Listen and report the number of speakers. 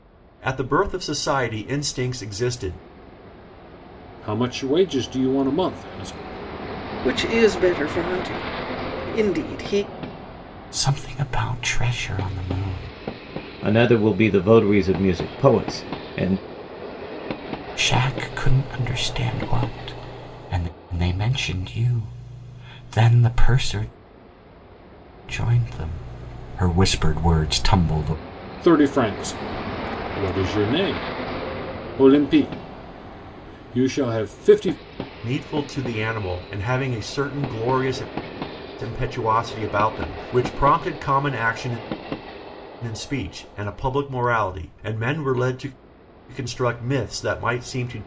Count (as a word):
five